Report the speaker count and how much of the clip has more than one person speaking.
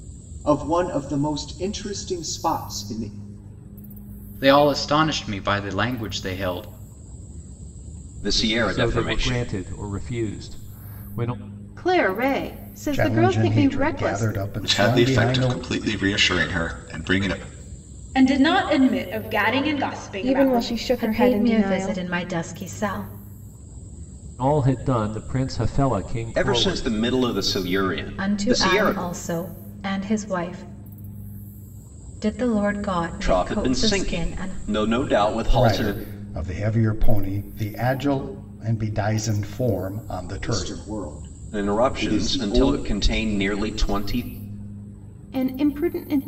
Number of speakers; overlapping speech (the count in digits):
10, about 22%